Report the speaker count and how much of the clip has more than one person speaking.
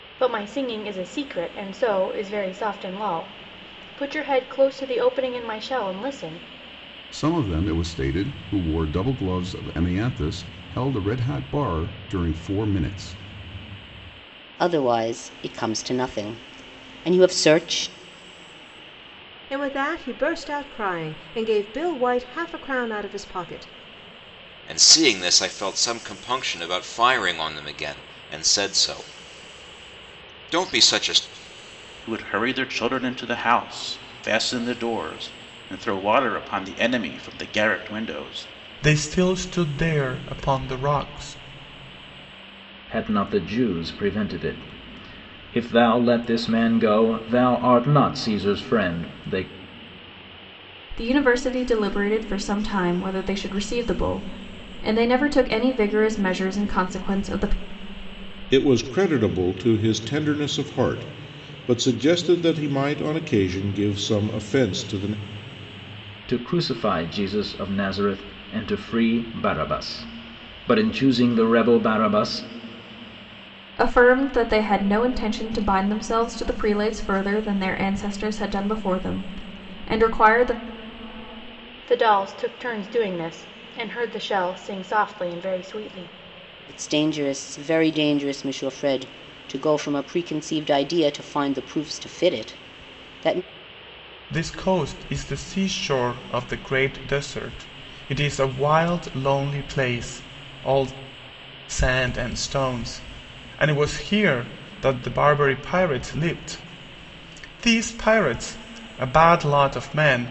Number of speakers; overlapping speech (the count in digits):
10, no overlap